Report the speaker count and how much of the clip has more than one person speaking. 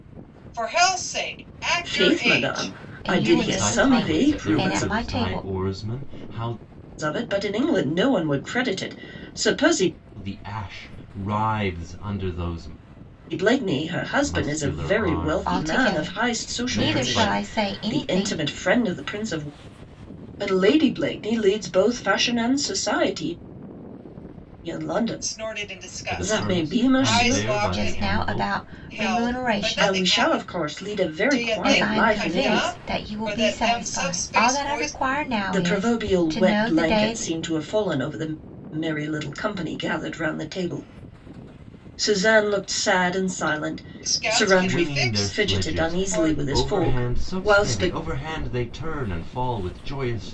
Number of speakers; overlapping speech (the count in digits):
4, about 46%